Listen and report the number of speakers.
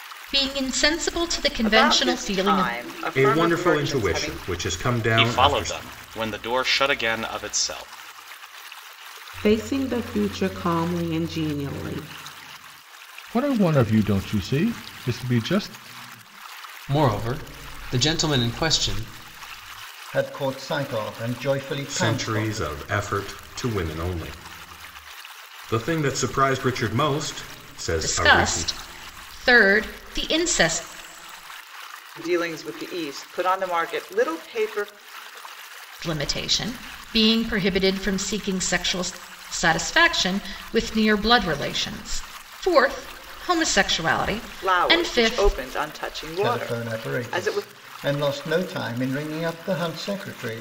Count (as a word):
eight